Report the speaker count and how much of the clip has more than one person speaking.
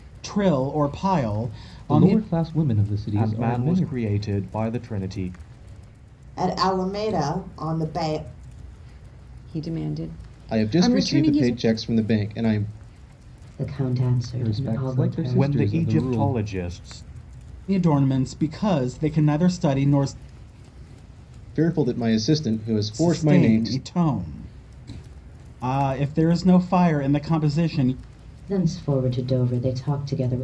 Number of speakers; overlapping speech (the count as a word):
seven, about 16%